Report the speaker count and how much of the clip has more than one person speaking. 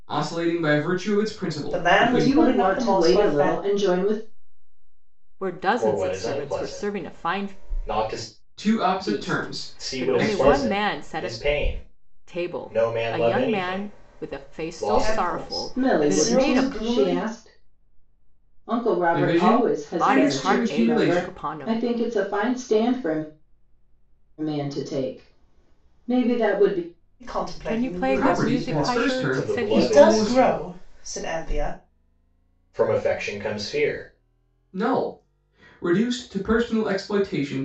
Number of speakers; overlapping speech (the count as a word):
five, about 44%